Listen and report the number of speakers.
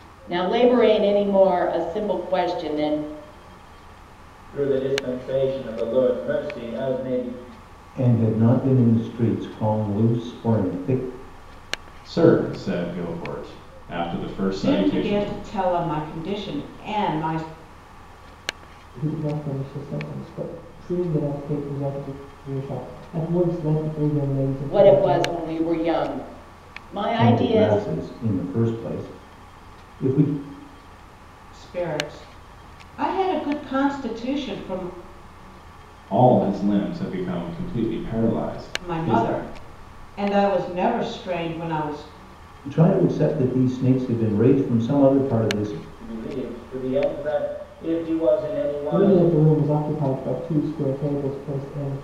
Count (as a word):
six